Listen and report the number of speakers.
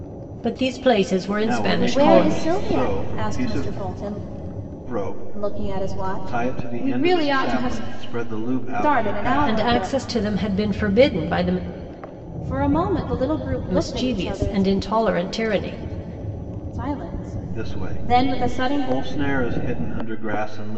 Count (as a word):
three